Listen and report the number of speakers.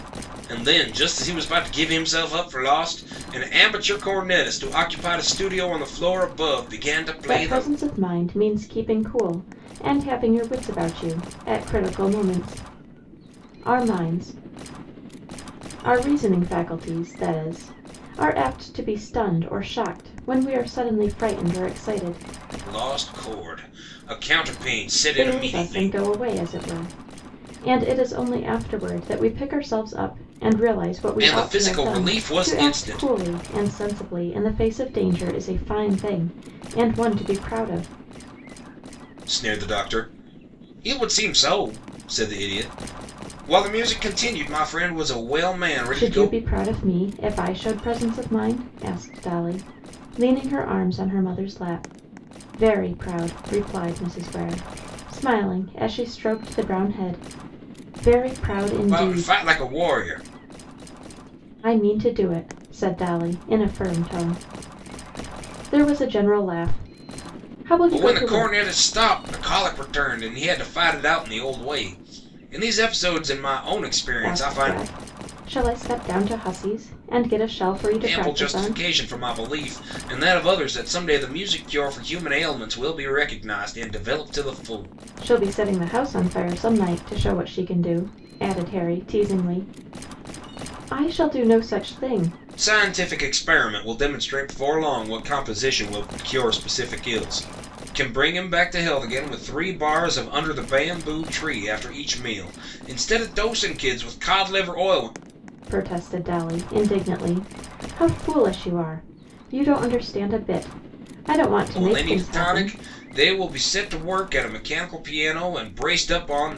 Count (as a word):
two